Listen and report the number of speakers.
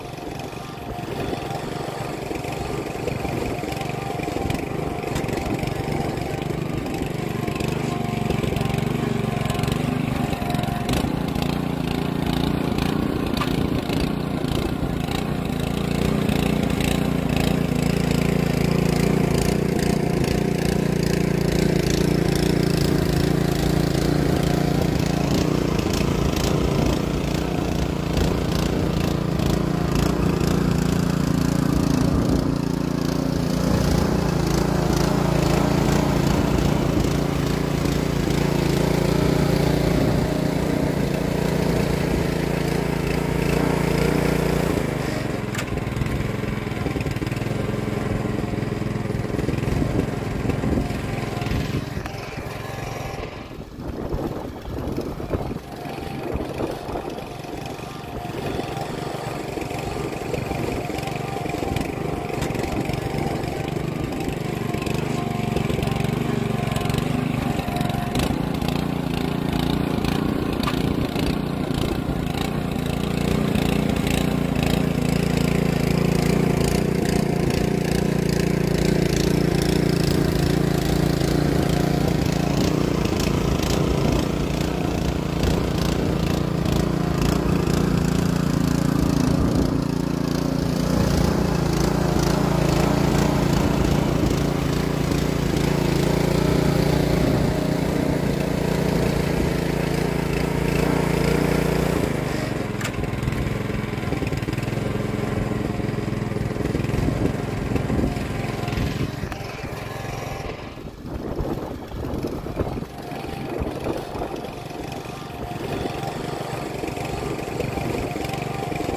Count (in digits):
0